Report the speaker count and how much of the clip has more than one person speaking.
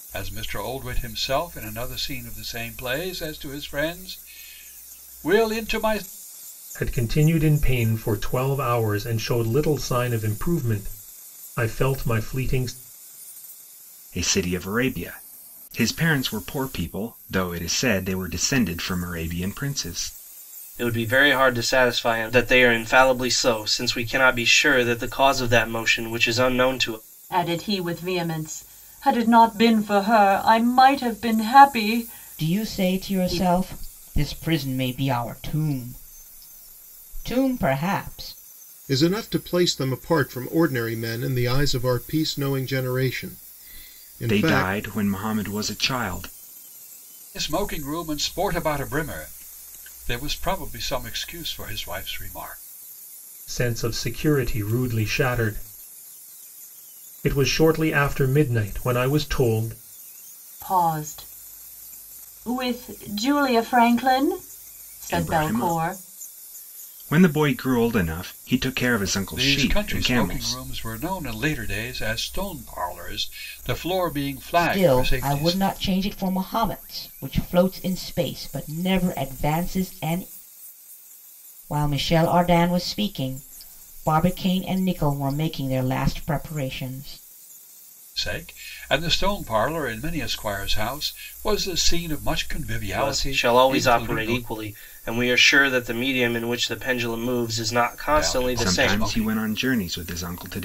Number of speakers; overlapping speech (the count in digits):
7, about 8%